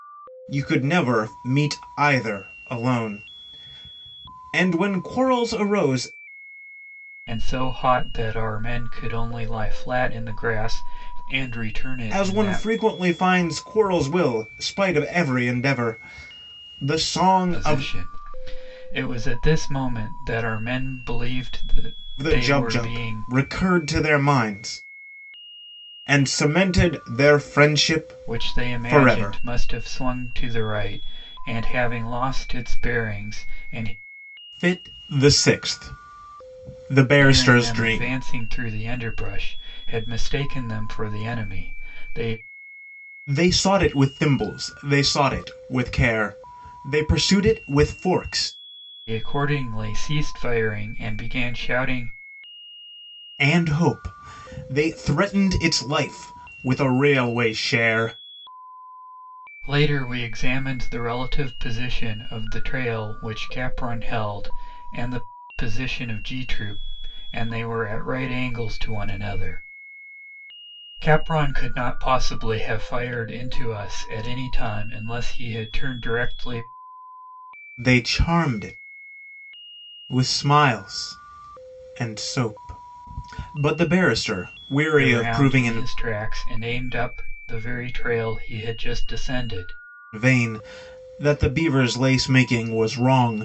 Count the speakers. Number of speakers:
2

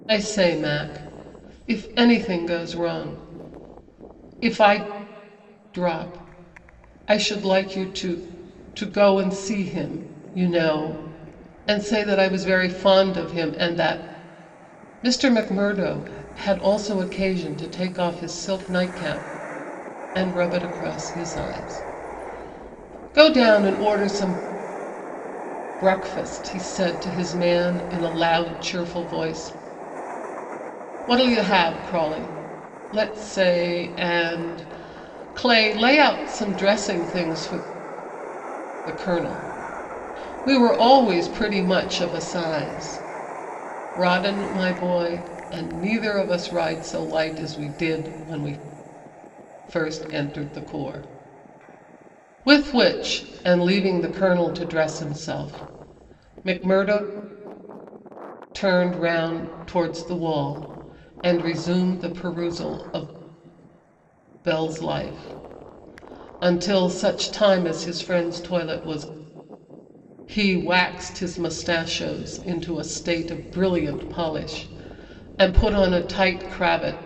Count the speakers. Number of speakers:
1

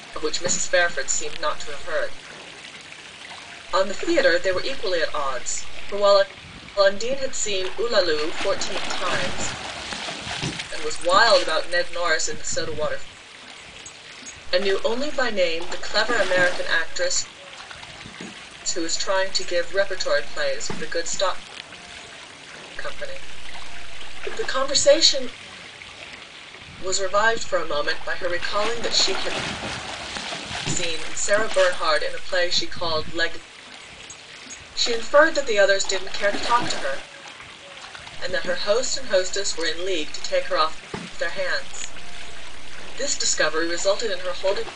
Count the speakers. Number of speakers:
1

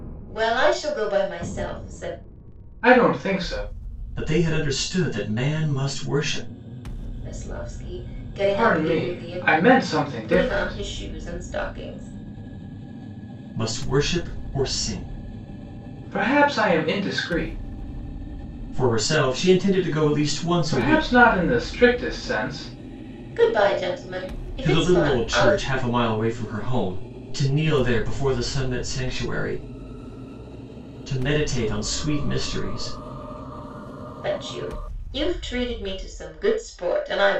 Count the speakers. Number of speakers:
3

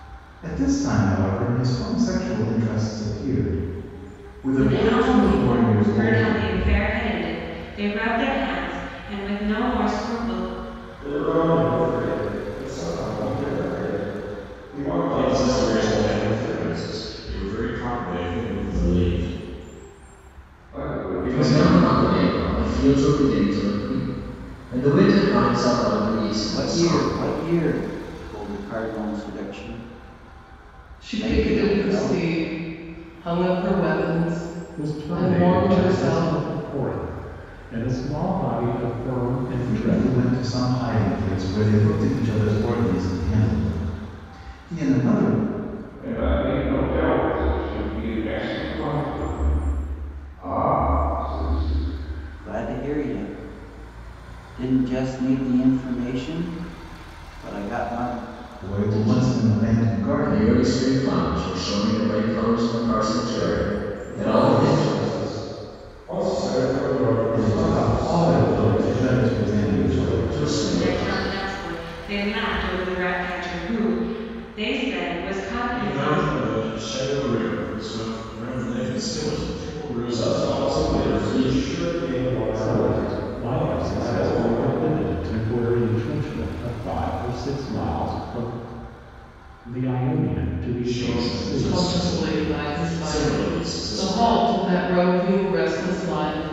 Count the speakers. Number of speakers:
9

